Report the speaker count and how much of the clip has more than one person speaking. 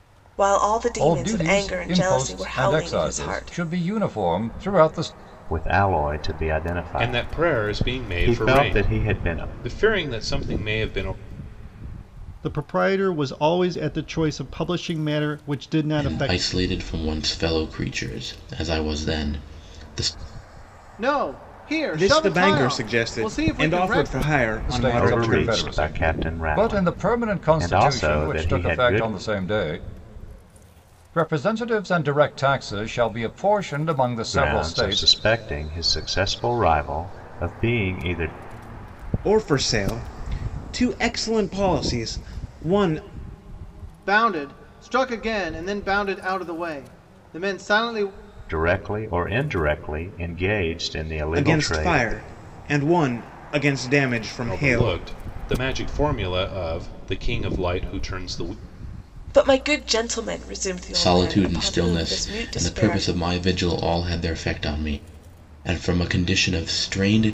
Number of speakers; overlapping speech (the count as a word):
eight, about 24%